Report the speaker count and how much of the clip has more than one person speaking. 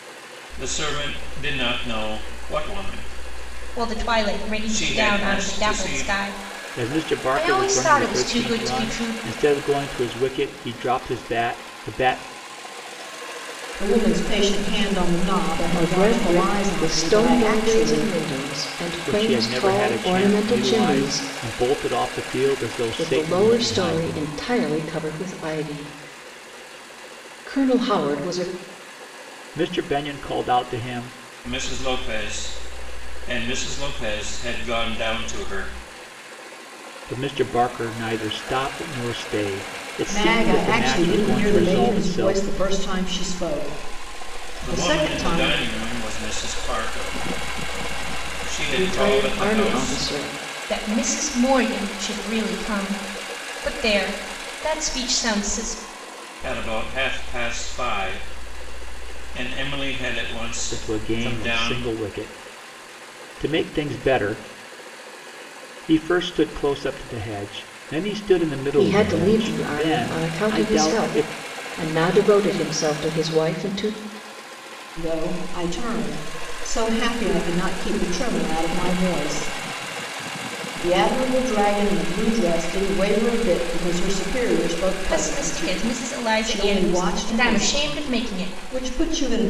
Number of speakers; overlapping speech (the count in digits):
5, about 25%